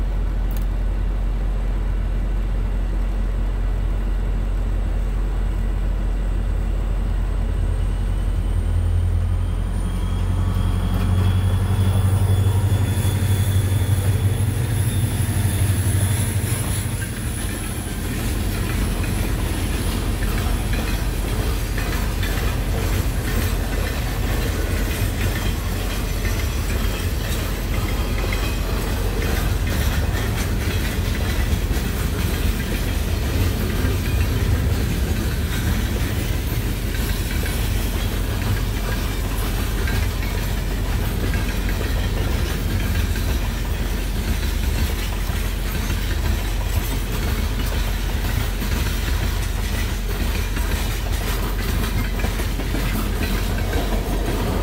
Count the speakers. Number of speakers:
0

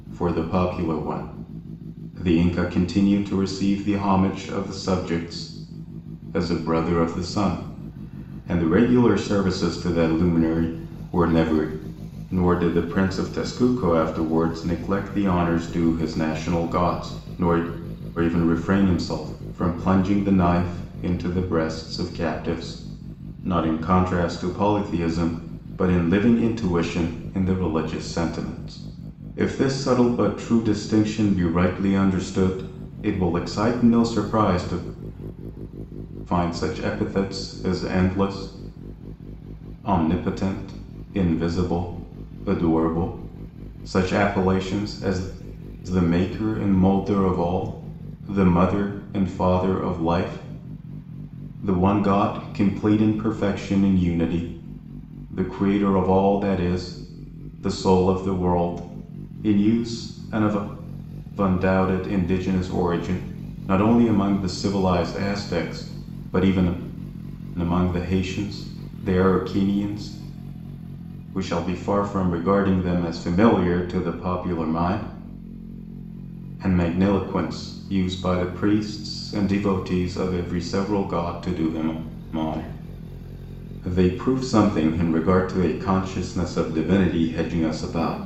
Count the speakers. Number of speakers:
1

